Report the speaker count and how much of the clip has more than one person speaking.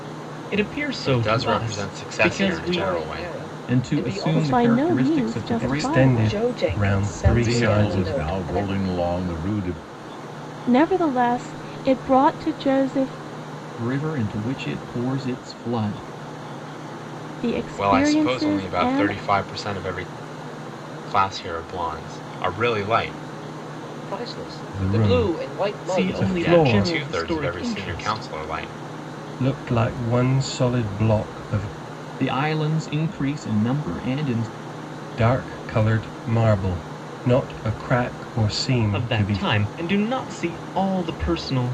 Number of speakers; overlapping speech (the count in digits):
8, about 31%